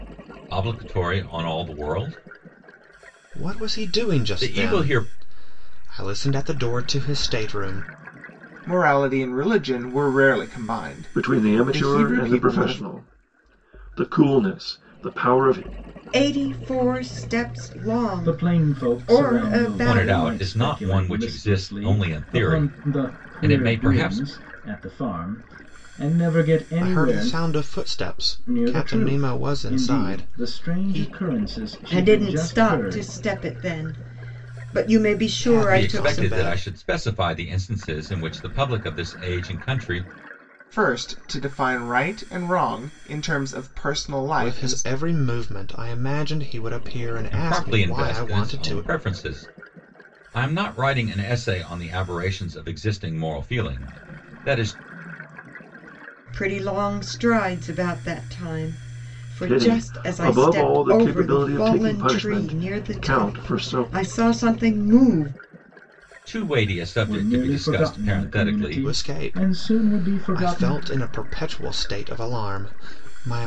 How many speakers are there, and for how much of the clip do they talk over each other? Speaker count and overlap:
six, about 35%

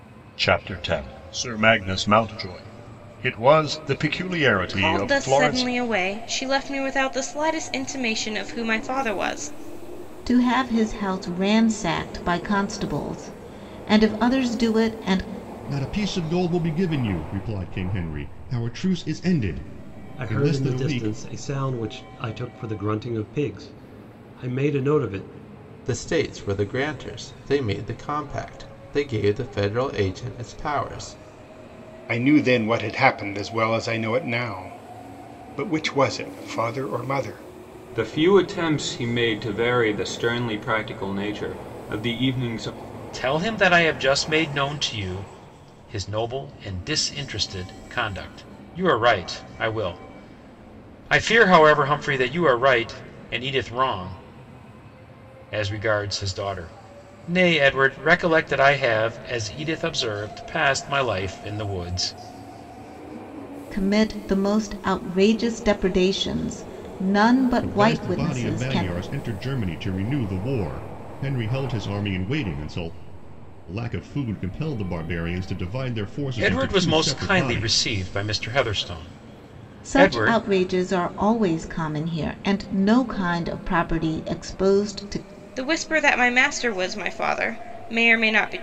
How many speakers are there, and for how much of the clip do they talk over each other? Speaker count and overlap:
nine, about 6%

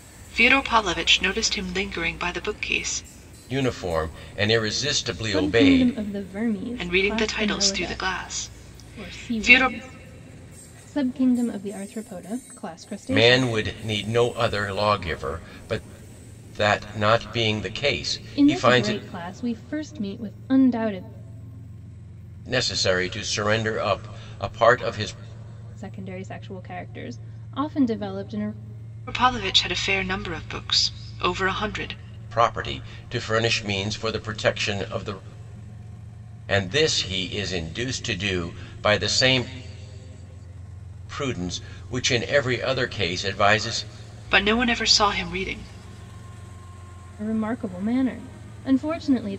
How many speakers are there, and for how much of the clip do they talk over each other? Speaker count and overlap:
three, about 8%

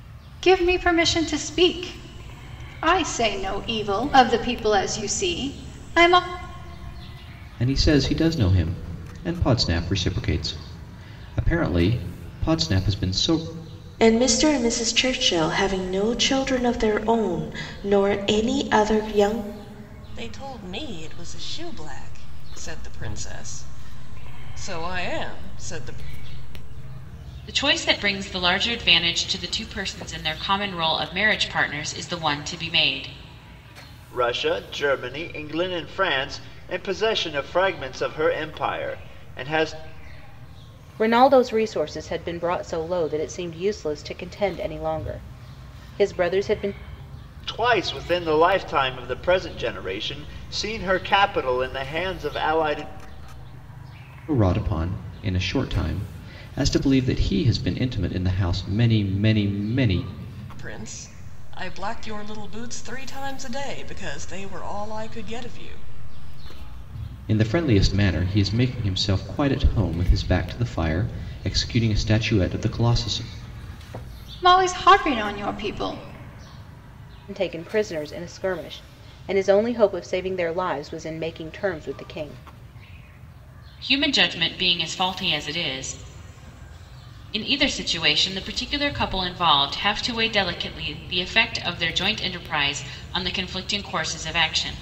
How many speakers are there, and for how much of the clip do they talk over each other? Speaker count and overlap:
seven, no overlap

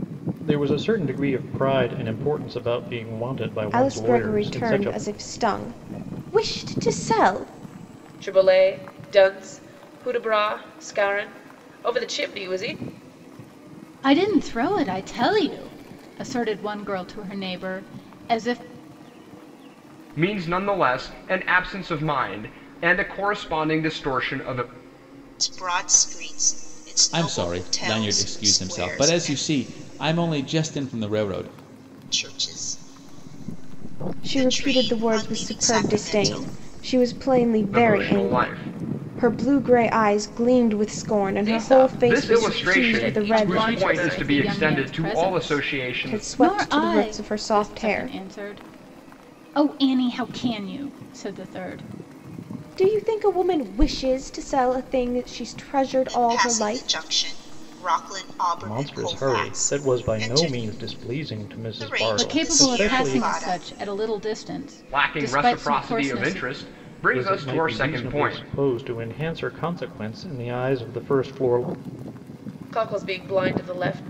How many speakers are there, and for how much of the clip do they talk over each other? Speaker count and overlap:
seven, about 29%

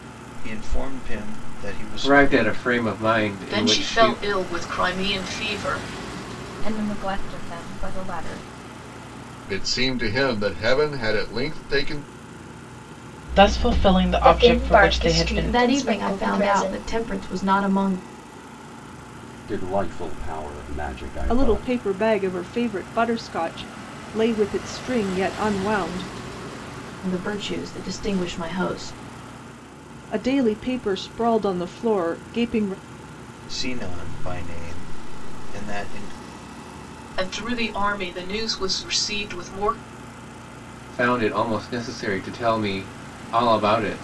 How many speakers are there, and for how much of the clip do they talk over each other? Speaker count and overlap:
ten, about 10%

